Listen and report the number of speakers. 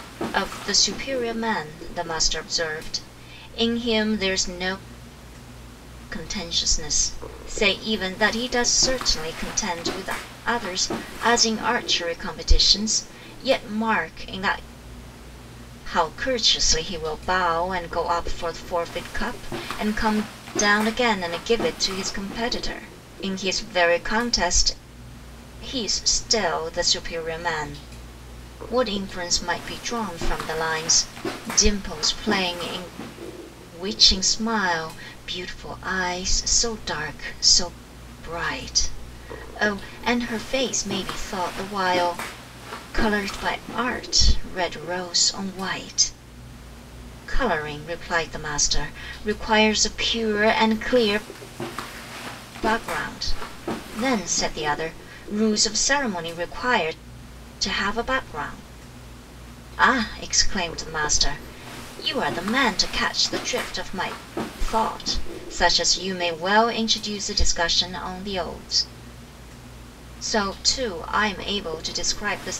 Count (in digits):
1